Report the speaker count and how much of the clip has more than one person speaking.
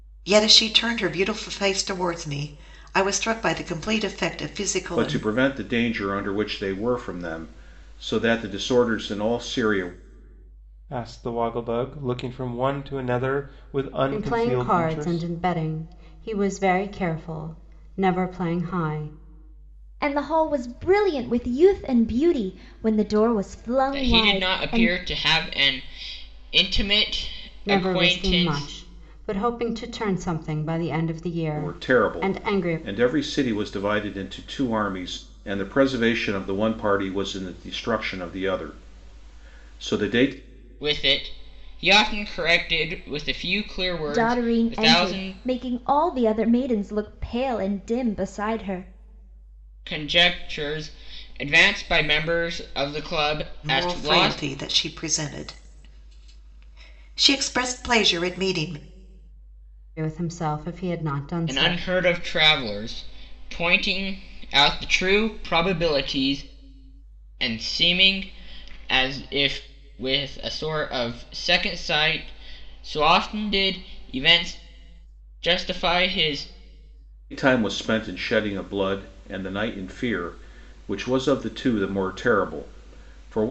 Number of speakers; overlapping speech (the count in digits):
6, about 9%